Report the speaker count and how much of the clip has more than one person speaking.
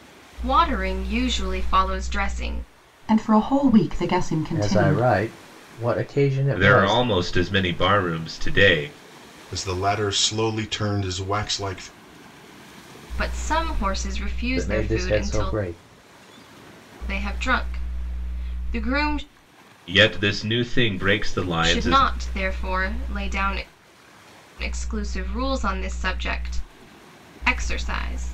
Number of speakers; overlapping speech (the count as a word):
five, about 9%